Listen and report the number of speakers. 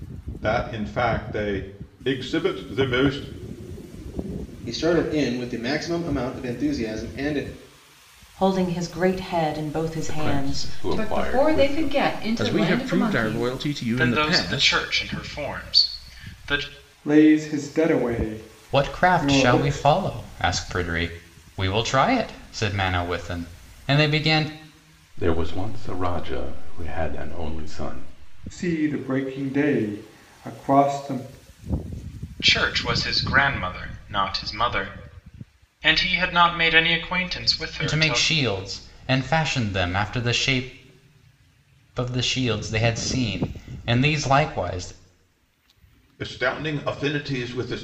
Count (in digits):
9